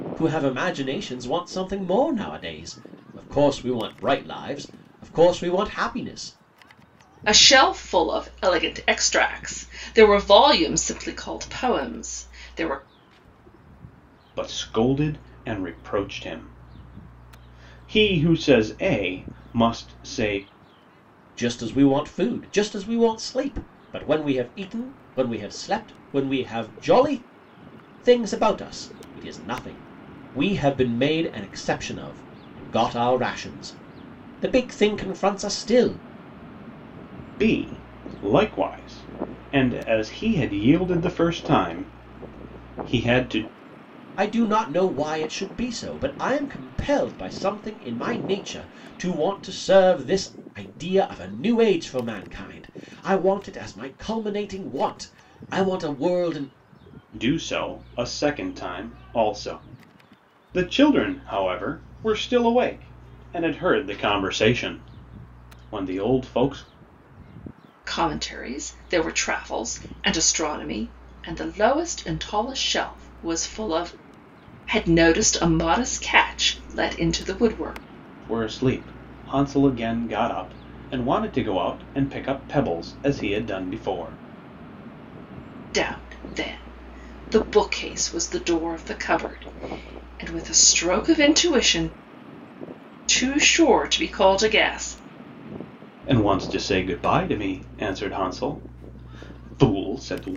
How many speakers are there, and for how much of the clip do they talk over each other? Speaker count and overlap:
3, no overlap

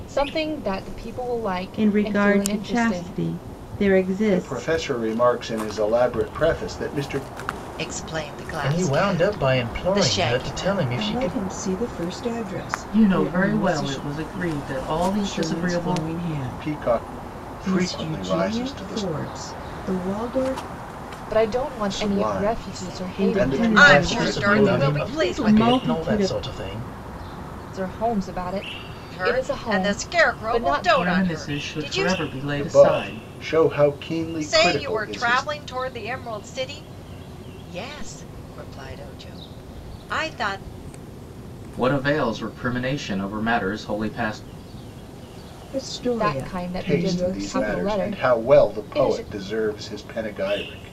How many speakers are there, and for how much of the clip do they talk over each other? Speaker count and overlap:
7, about 42%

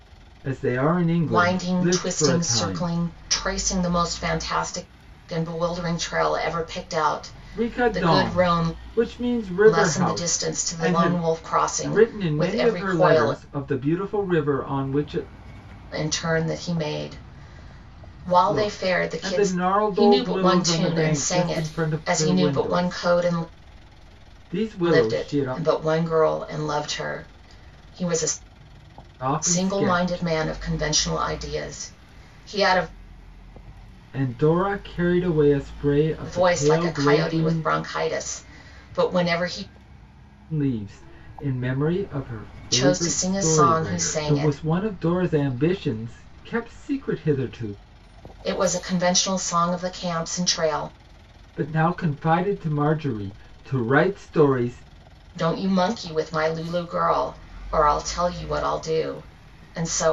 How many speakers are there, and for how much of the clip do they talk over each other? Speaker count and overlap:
2, about 26%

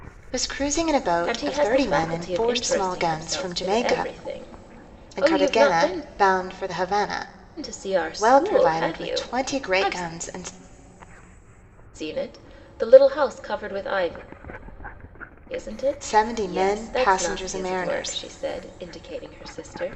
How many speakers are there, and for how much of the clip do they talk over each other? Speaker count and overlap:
2, about 40%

